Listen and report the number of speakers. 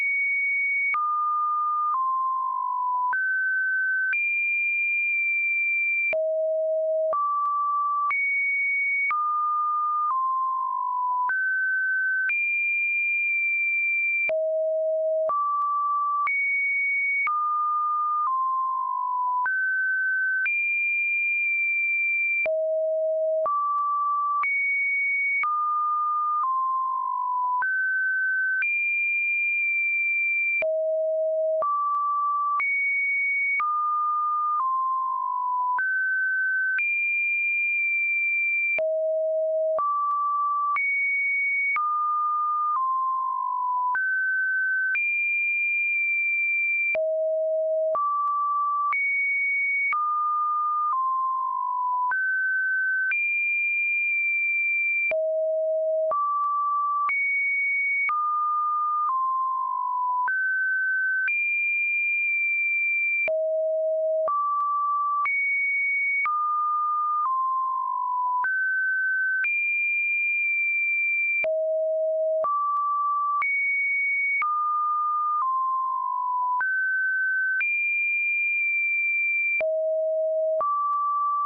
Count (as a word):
zero